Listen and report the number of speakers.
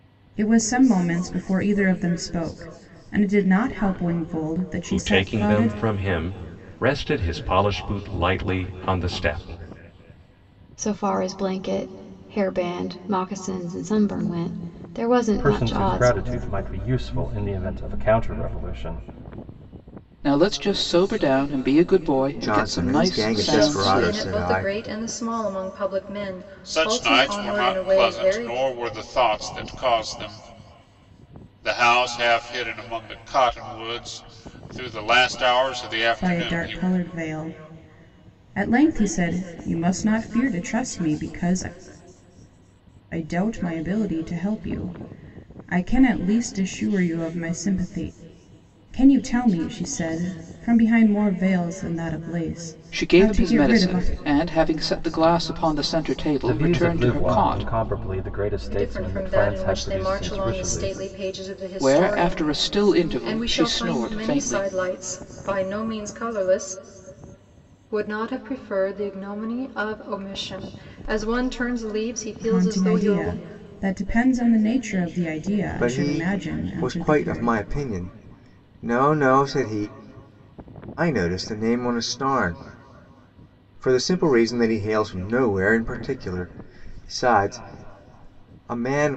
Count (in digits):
8